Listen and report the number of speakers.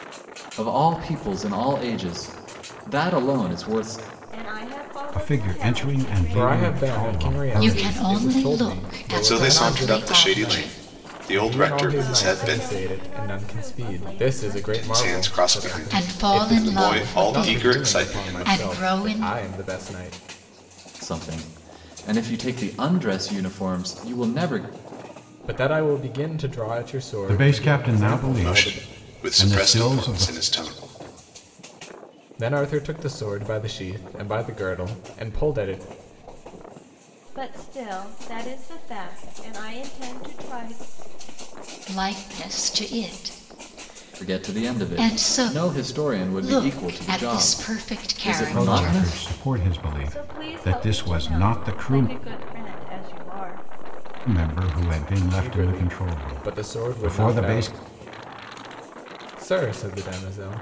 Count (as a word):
six